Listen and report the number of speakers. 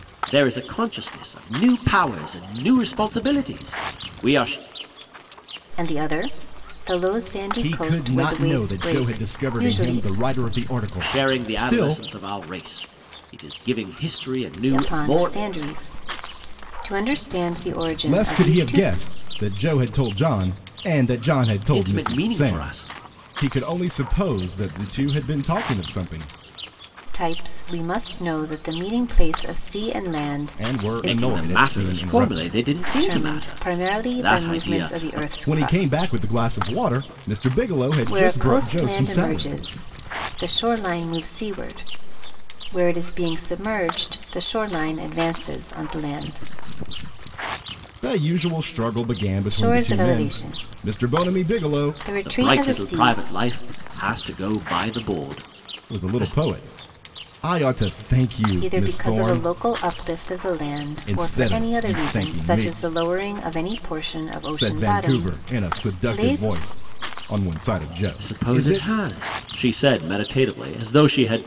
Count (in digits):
3